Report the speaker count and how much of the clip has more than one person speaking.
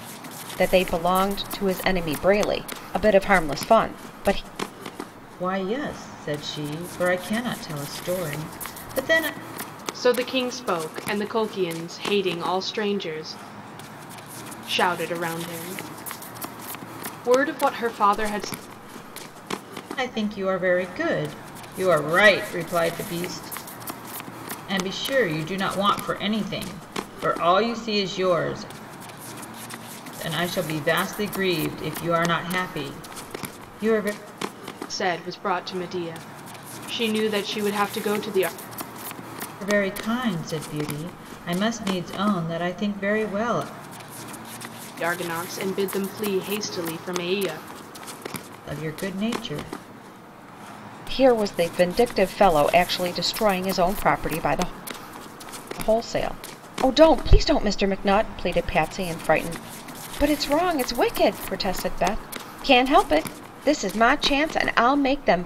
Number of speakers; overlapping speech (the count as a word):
three, no overlap